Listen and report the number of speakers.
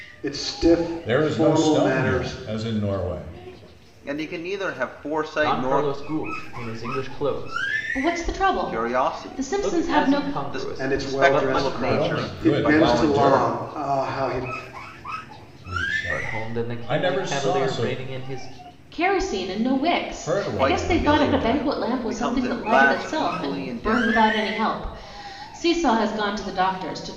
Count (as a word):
five